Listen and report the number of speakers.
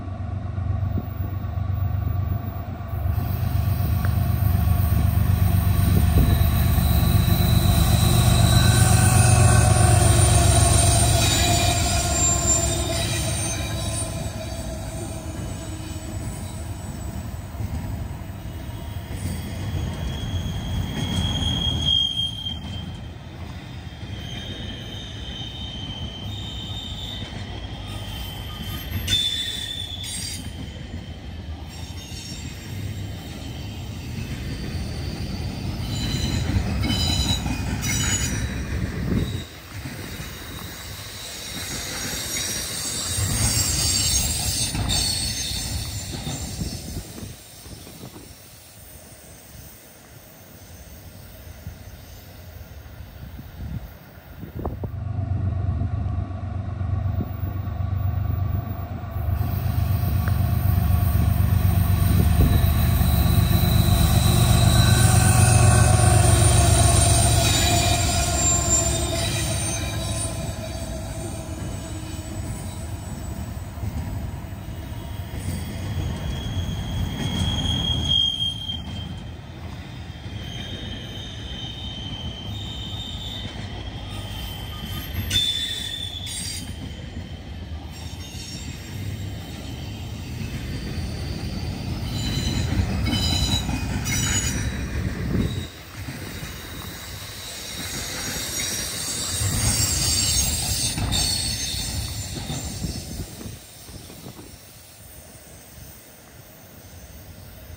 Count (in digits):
0